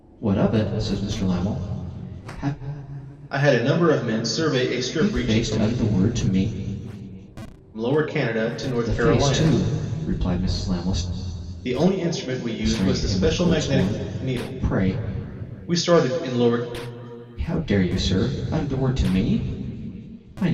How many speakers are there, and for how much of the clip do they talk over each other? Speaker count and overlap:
two, about 18%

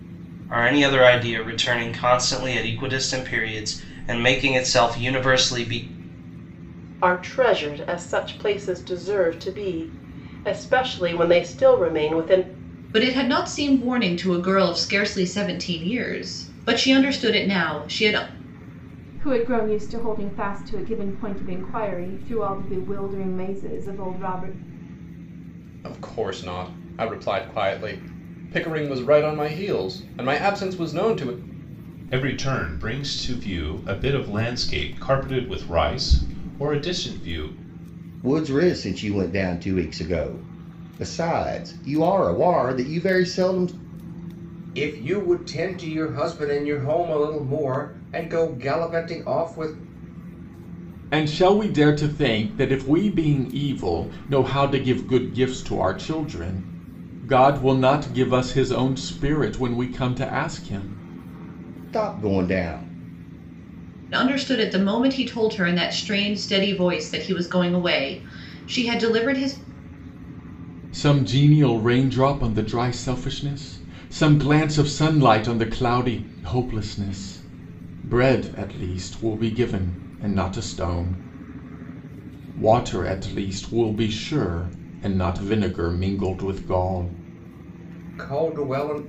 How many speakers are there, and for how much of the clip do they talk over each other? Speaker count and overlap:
nine, no overlap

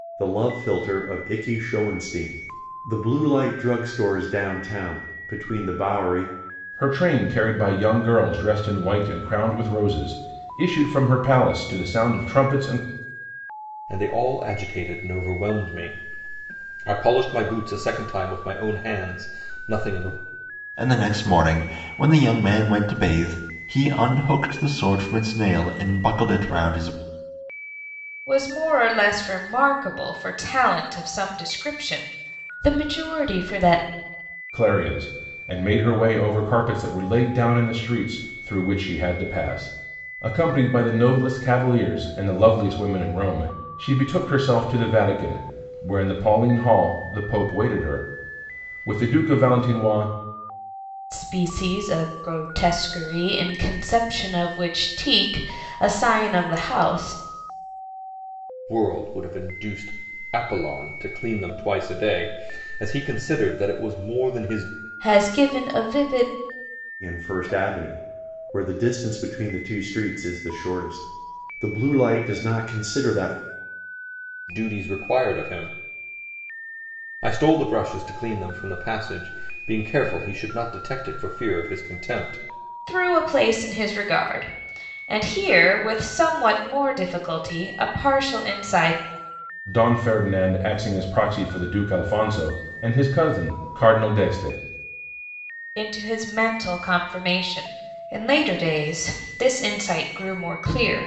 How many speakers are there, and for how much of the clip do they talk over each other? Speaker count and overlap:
five, no overlap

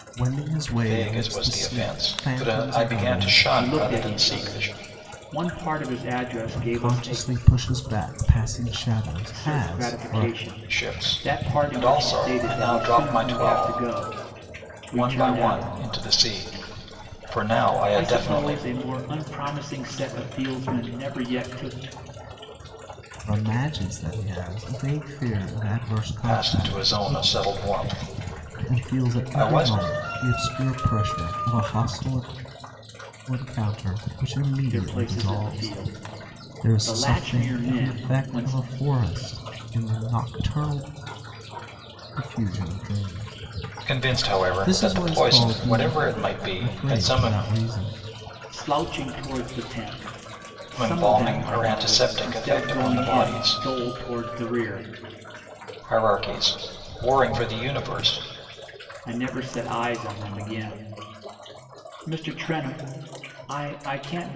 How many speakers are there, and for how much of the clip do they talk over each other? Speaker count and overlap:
three, about 34%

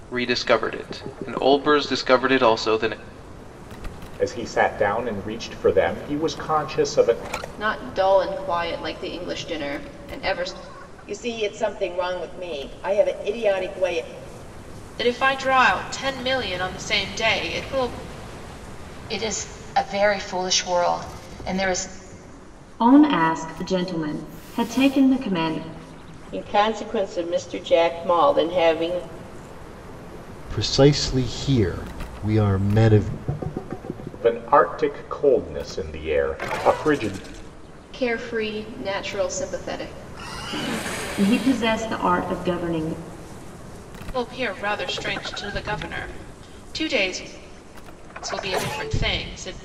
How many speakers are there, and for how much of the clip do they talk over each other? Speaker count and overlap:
nine, no overlap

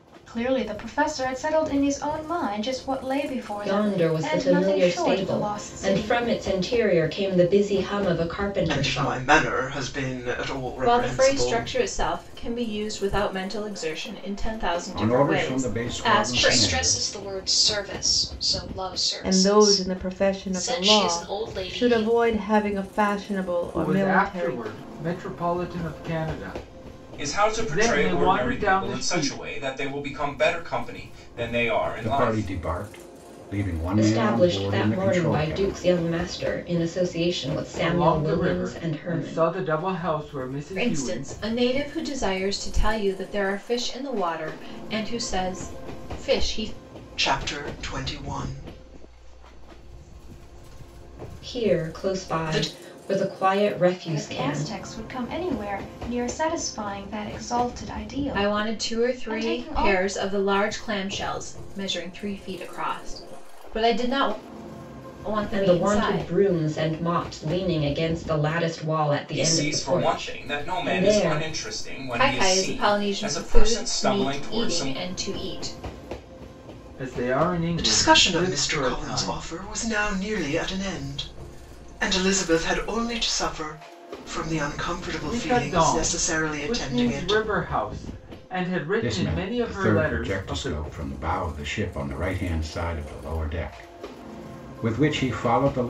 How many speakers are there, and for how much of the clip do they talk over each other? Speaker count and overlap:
nine, about 34%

